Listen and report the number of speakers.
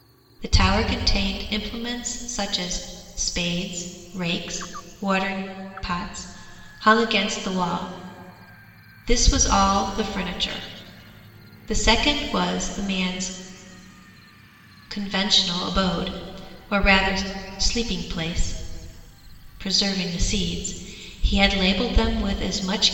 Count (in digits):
1